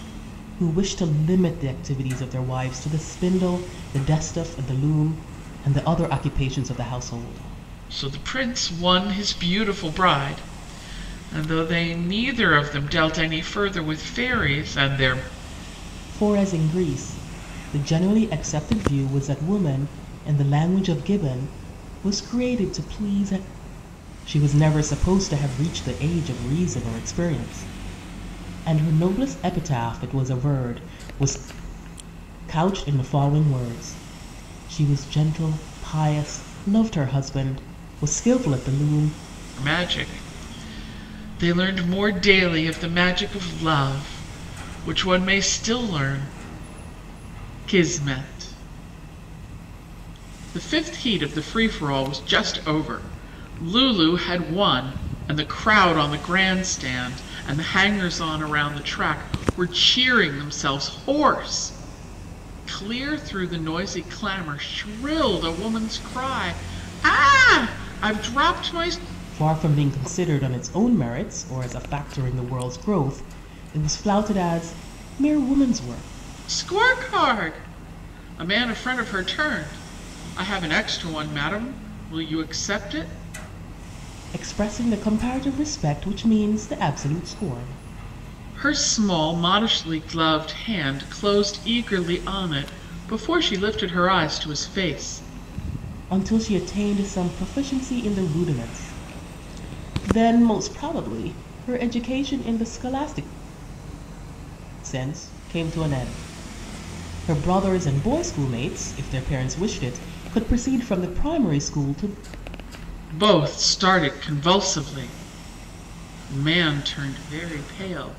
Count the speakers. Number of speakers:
2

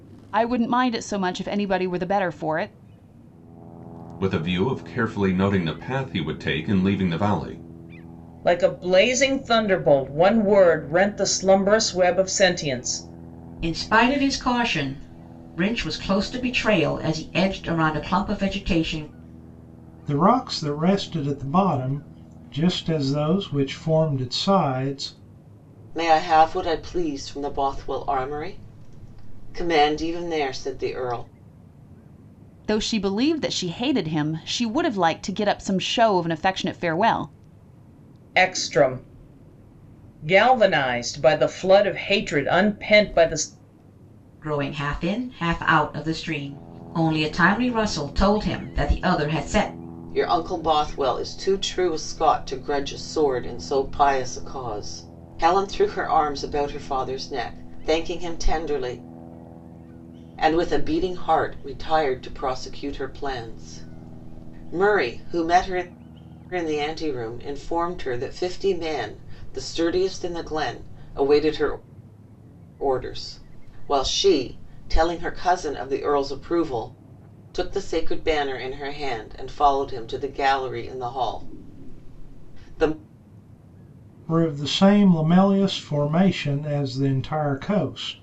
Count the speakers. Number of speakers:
6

